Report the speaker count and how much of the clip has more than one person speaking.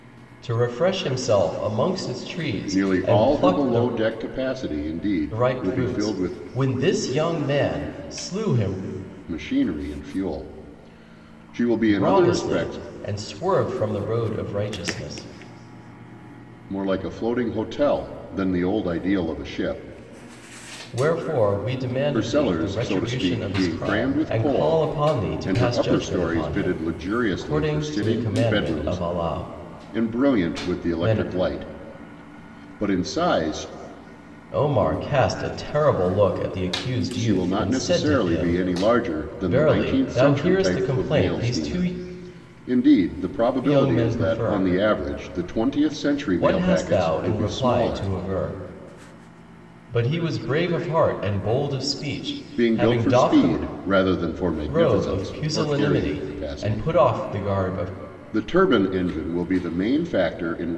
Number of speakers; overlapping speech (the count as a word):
two, about 38%